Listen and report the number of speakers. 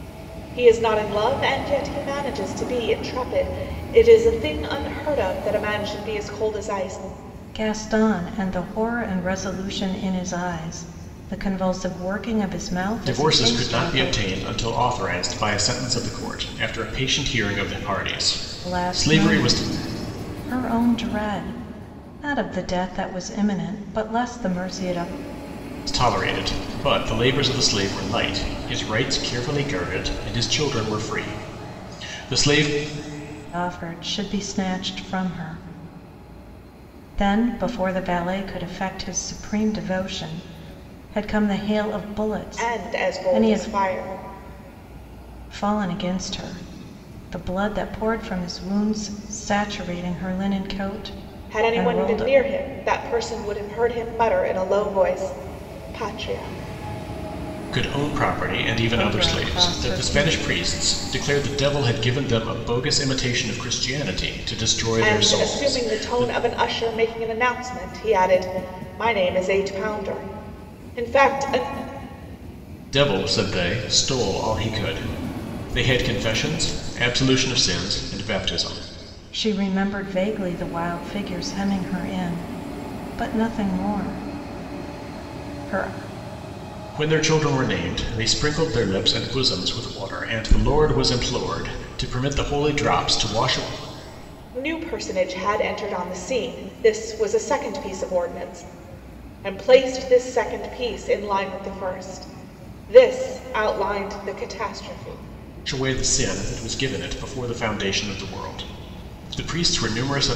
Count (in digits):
3